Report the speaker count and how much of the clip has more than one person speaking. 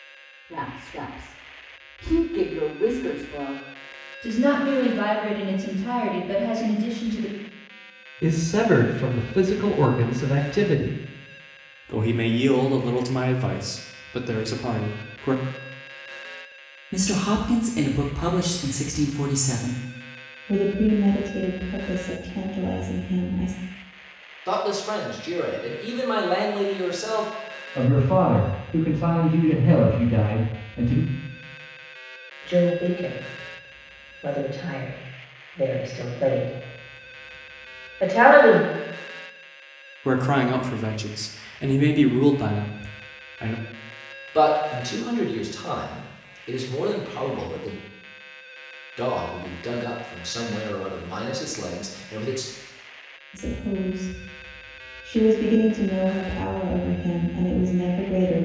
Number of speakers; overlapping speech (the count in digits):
9, no overlap